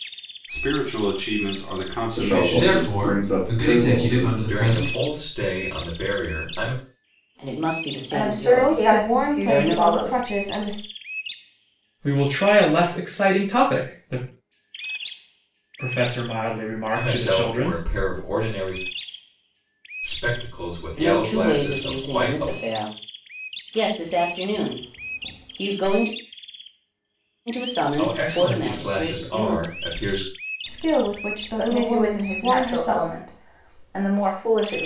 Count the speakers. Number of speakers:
8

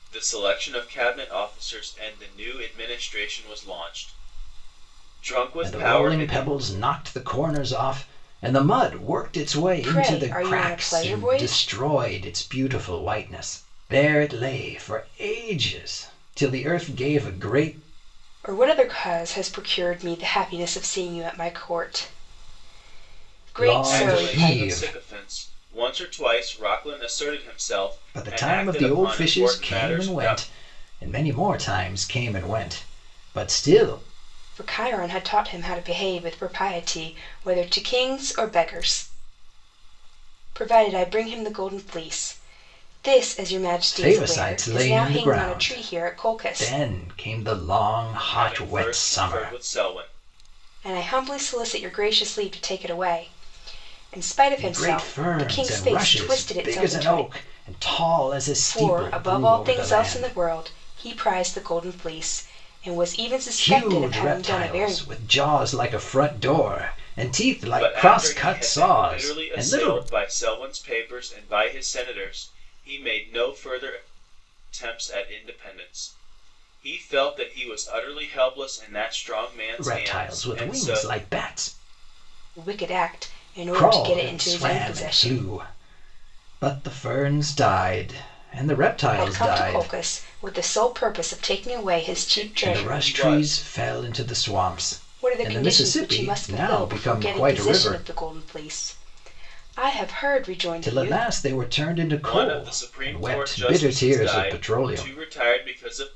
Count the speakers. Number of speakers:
3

